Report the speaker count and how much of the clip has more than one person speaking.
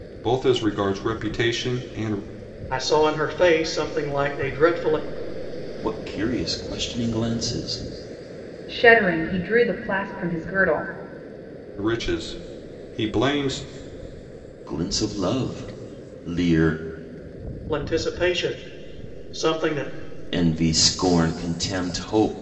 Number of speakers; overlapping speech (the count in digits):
4, no overlap